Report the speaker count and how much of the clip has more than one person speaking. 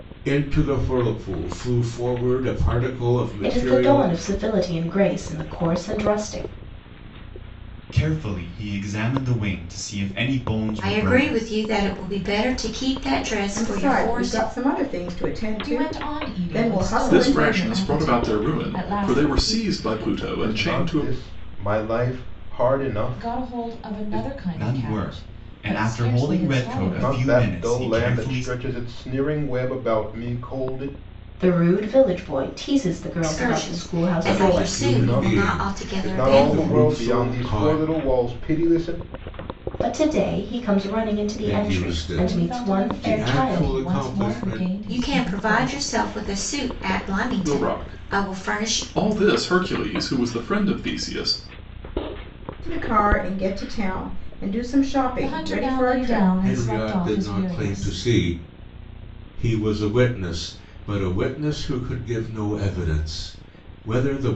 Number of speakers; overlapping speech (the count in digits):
8, about 40%